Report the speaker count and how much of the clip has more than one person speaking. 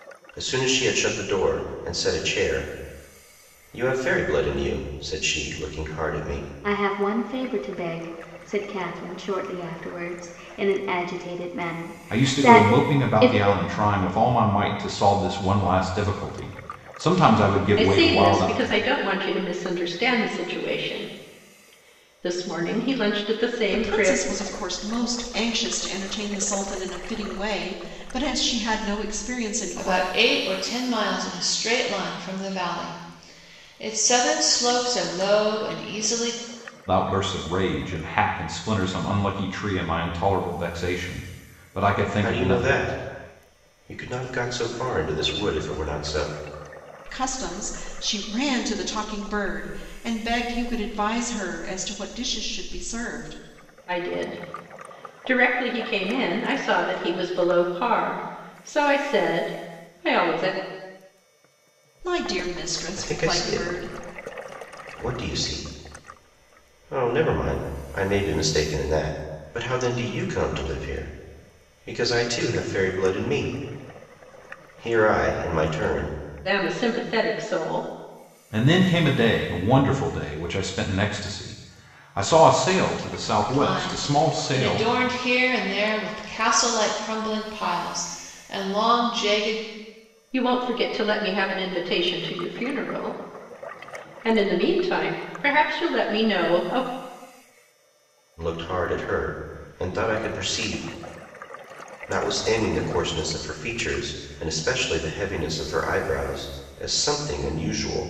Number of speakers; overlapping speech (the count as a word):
six, about 6%